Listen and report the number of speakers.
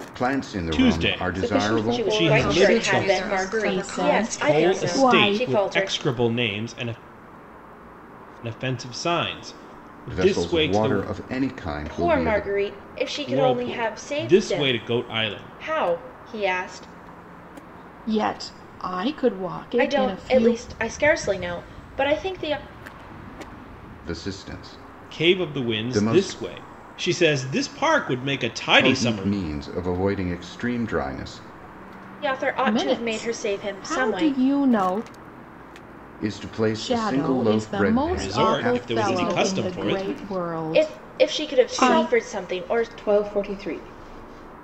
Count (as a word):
six